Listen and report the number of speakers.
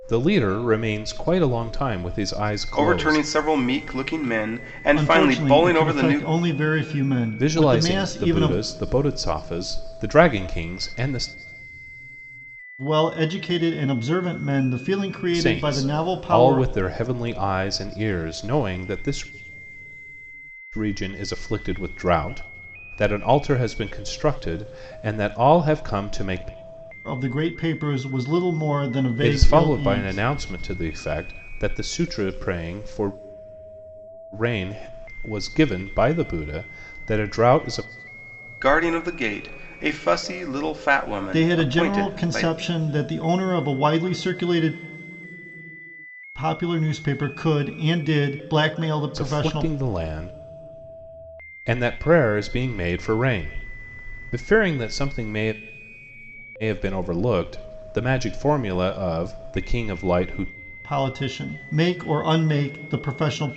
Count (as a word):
three